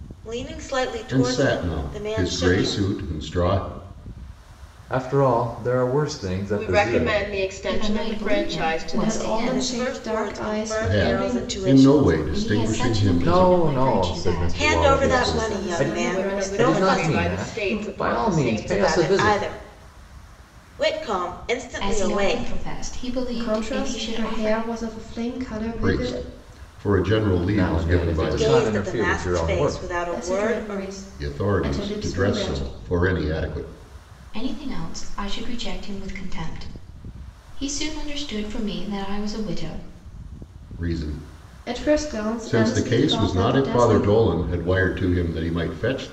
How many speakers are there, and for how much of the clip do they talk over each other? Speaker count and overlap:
6, about 52%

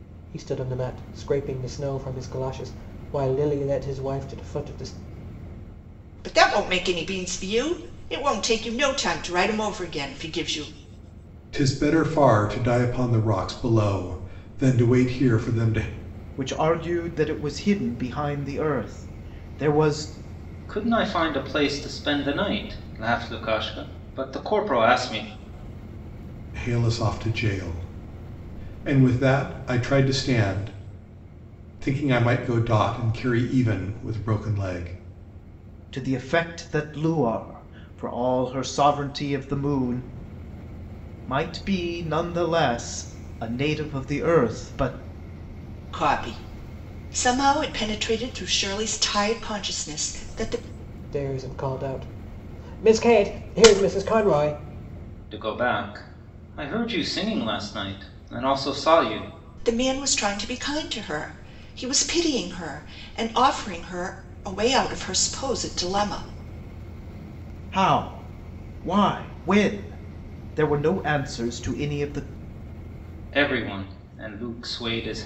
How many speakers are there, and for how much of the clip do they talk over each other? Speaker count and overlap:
5, no overlap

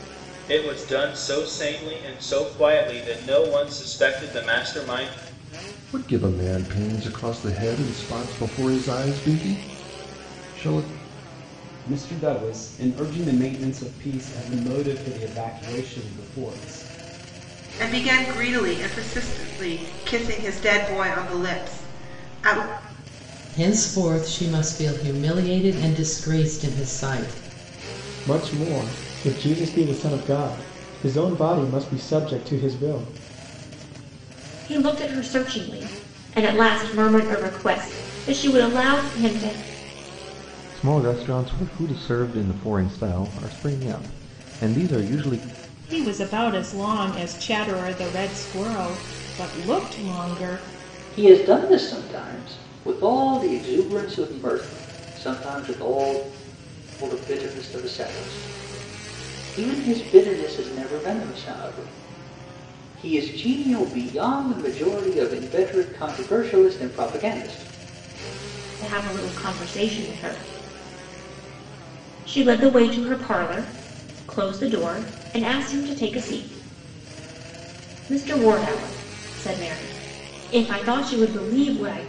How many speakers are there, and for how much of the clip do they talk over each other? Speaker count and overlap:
10, no overlap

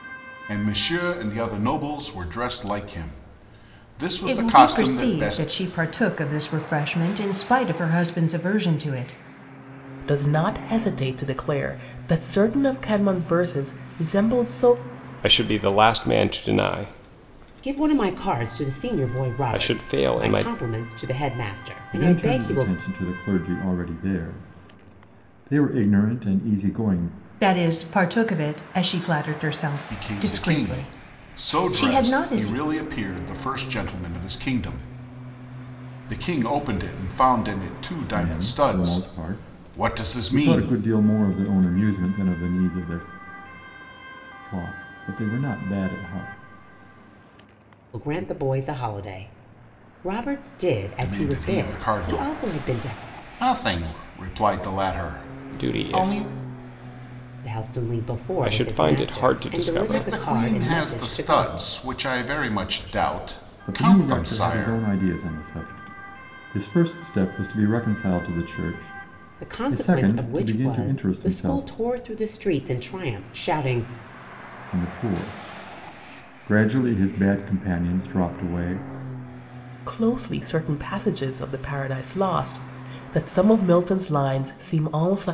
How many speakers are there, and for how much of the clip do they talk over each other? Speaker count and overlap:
6, about 25%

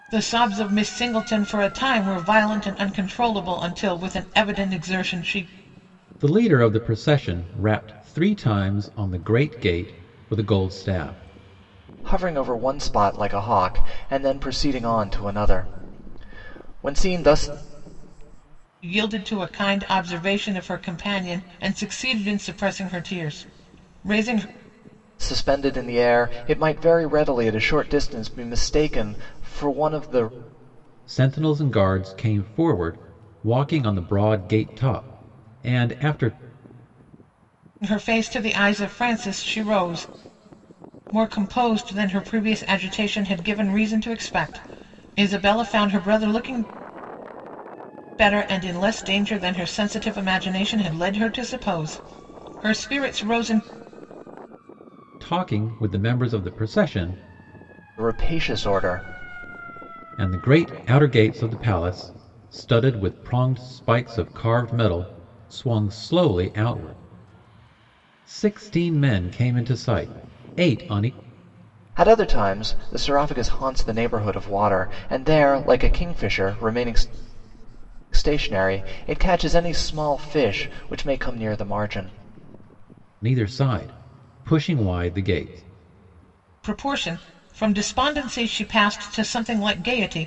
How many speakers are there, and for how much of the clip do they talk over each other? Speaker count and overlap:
3, no overlap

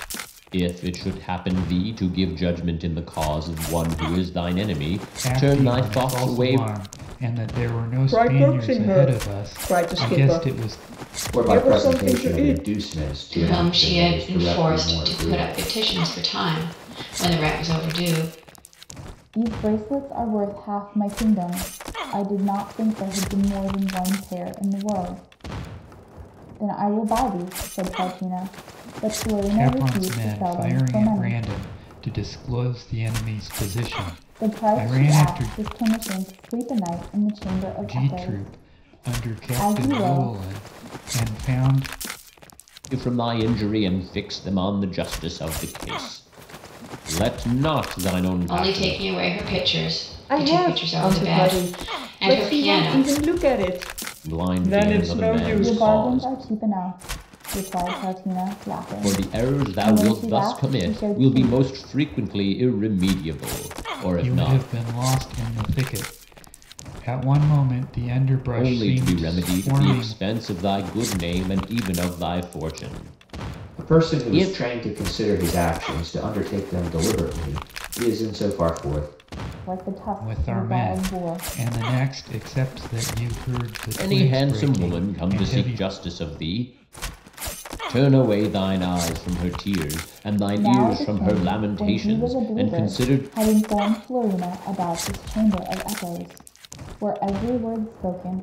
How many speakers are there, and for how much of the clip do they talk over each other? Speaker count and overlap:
6, about 31%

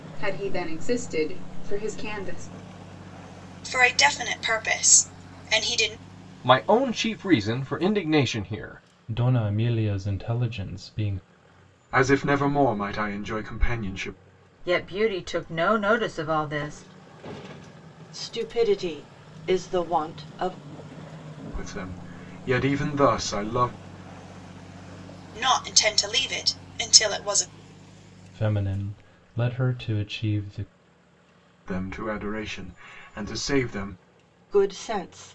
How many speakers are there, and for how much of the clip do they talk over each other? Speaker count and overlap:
7, no overlap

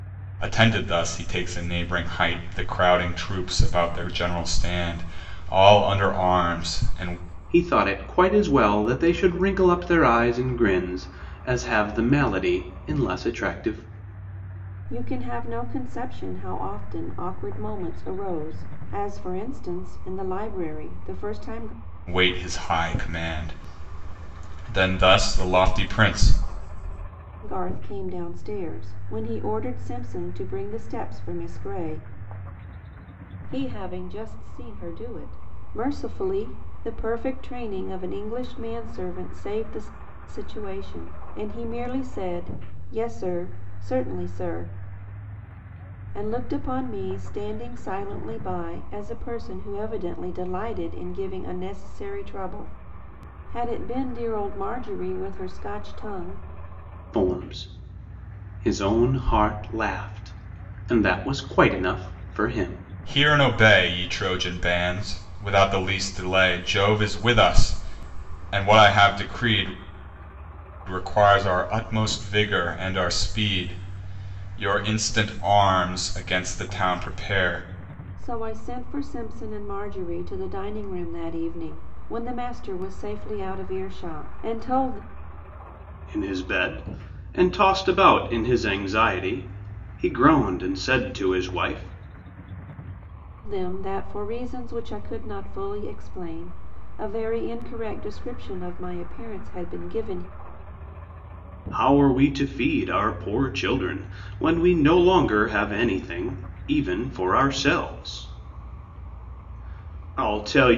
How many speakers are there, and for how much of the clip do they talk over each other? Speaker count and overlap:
3, no overlap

